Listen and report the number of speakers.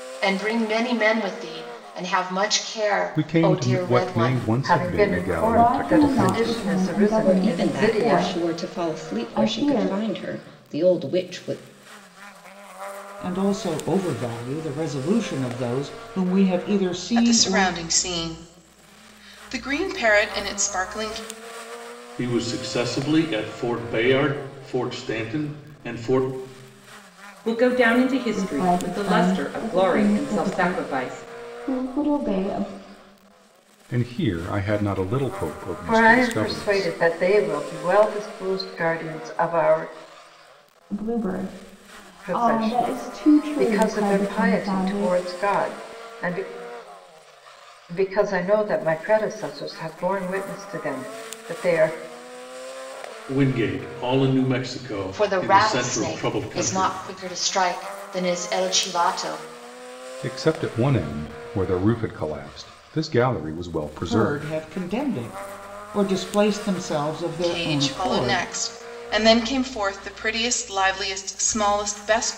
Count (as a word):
nine